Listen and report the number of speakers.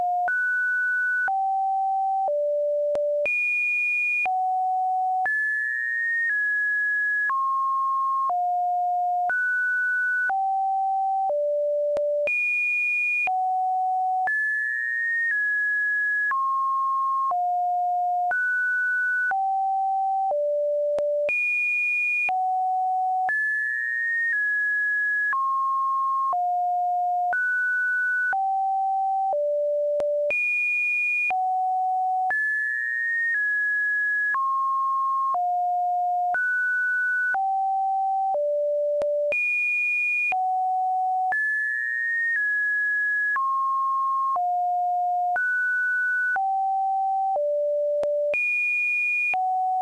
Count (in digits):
0